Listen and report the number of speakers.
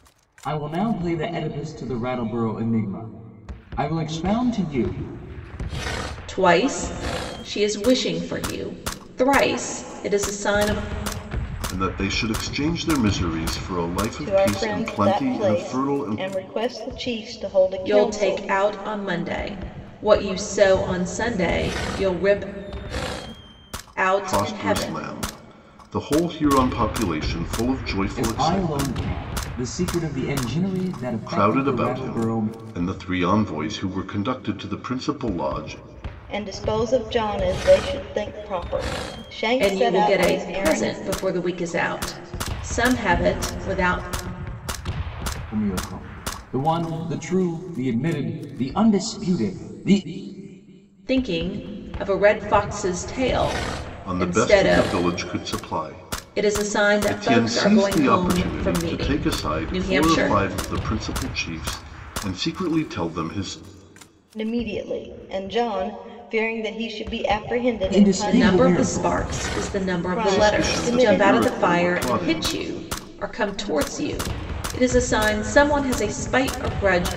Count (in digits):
4